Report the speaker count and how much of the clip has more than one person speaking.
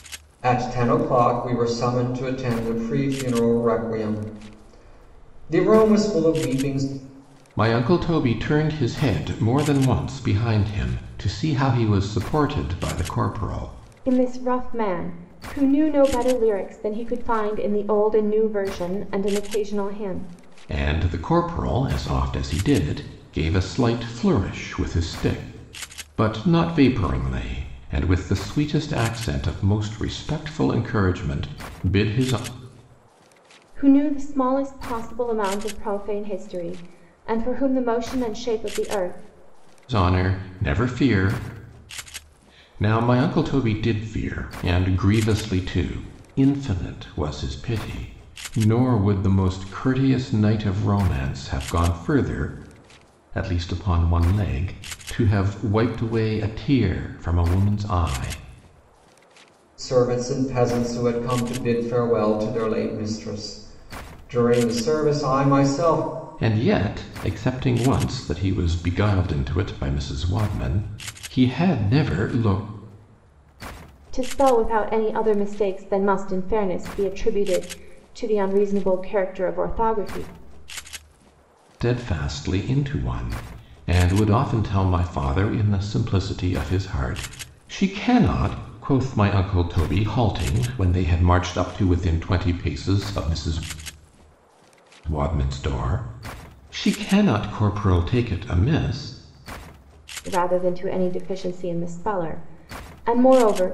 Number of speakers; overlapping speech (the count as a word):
three, no overlap